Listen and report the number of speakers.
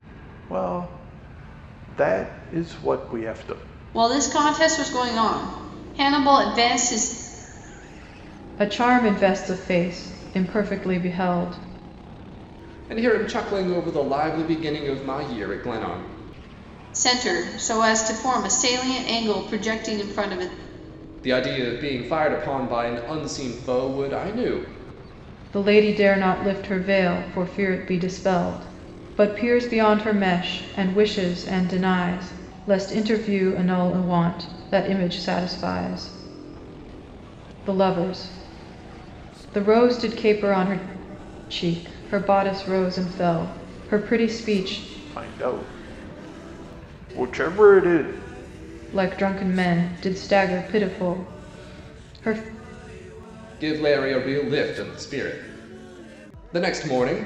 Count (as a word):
four